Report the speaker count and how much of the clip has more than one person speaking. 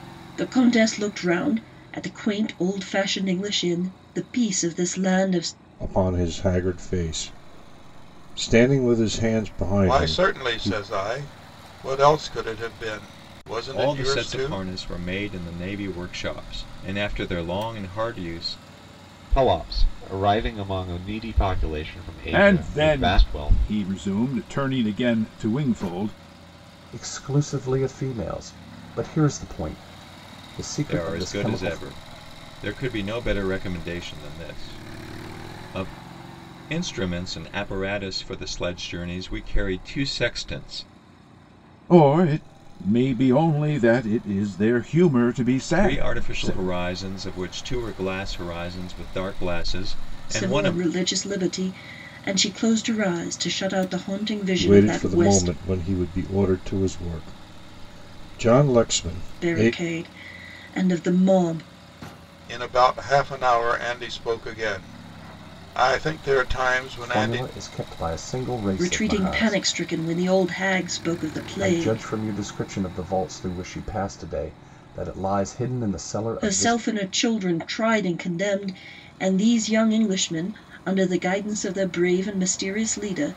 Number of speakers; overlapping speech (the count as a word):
seven, about 11%